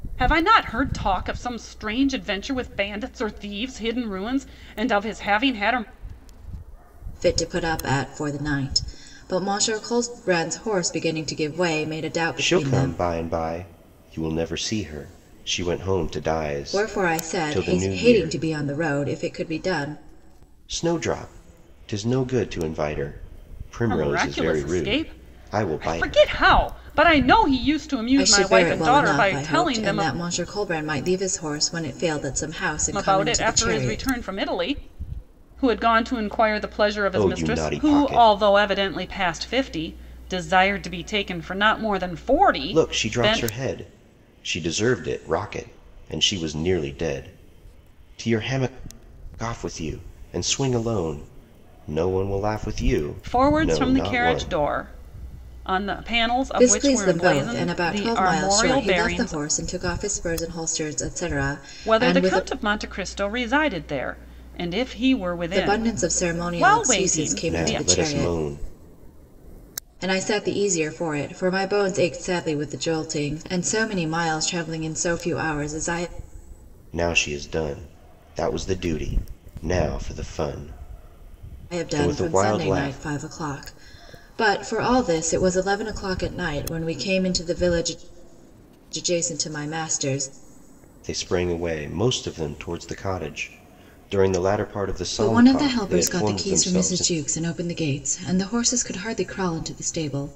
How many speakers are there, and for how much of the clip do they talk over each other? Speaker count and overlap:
3, about 21%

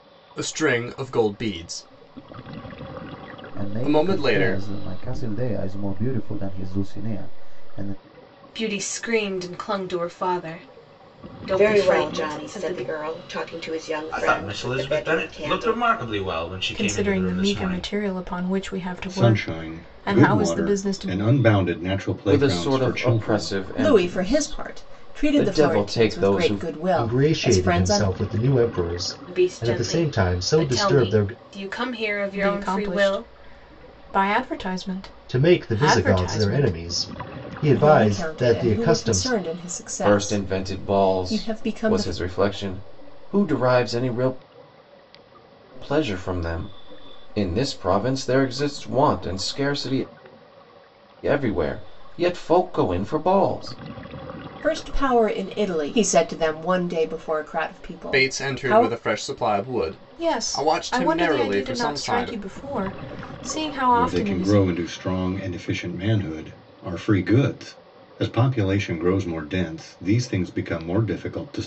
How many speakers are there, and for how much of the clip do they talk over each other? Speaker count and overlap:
10, about 35%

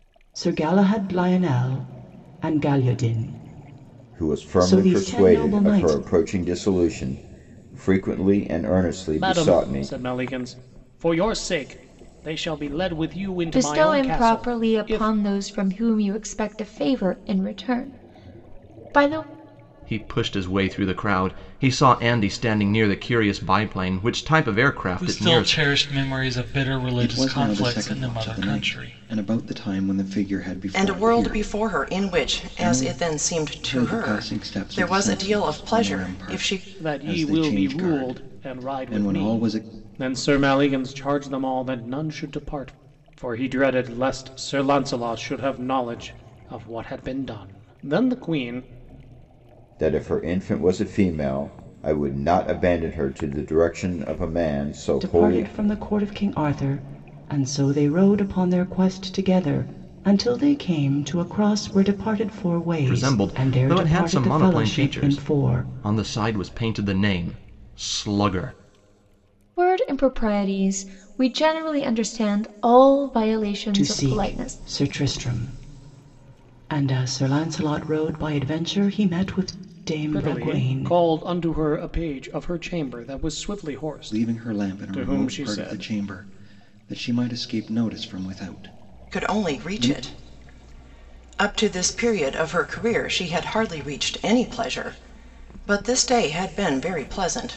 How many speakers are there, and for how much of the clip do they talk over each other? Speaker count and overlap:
8, about 24%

